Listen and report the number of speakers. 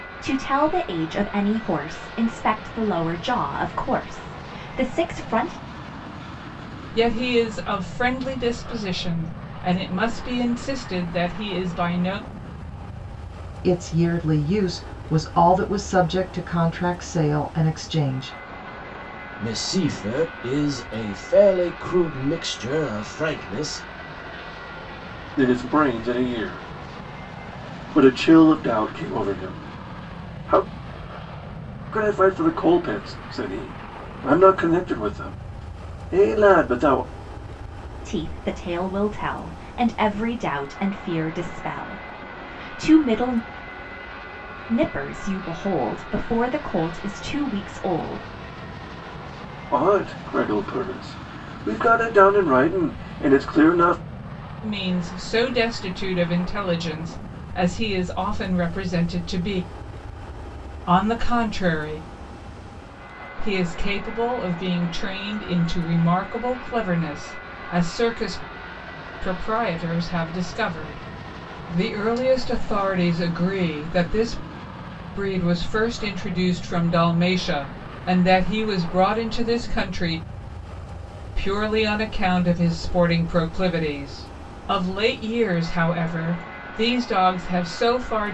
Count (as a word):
five